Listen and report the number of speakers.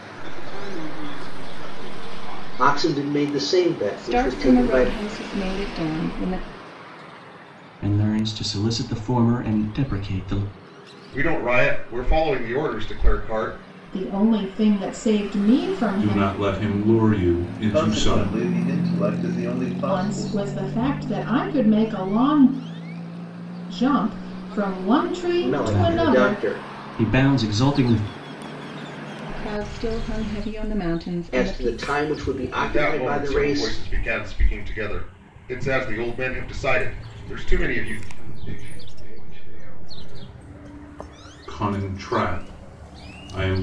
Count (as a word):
eight